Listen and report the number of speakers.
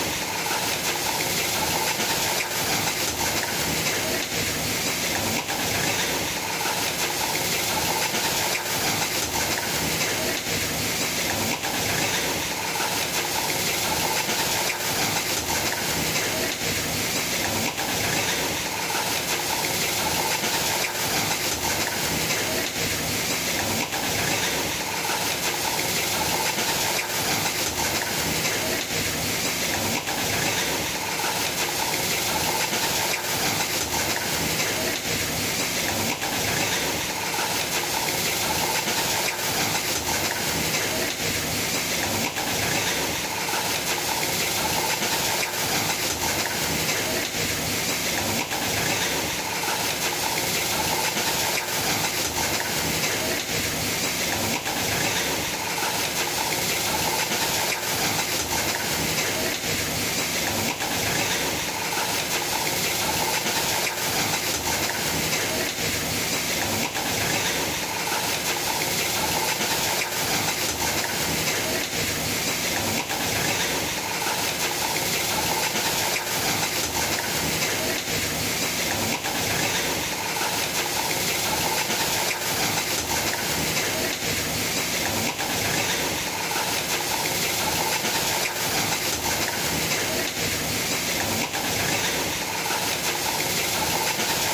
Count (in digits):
0